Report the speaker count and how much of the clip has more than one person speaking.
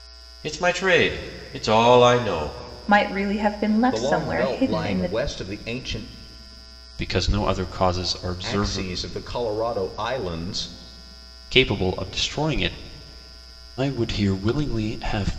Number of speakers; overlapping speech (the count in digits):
4, about 12%